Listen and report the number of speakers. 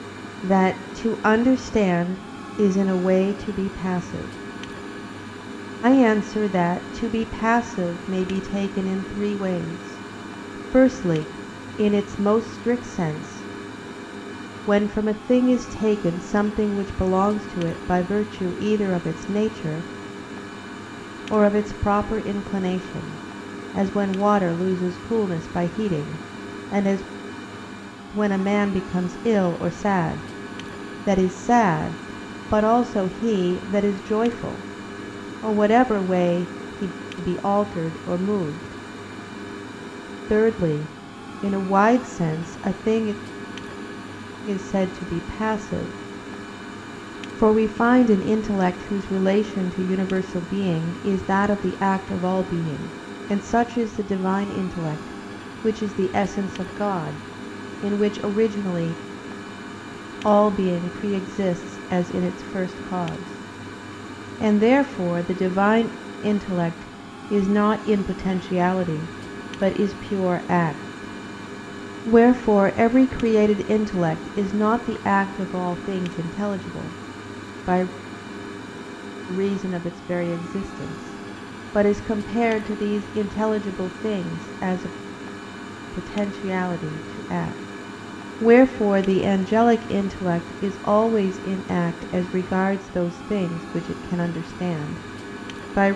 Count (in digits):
1